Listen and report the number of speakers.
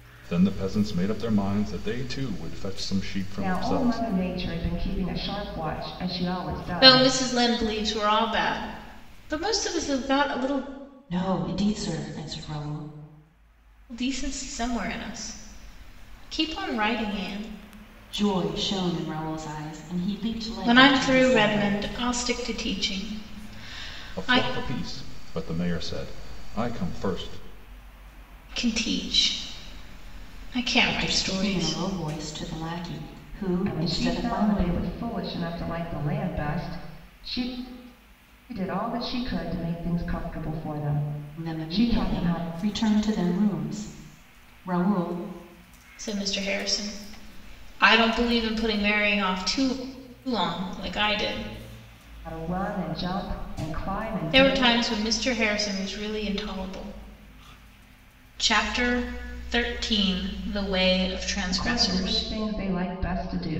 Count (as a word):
four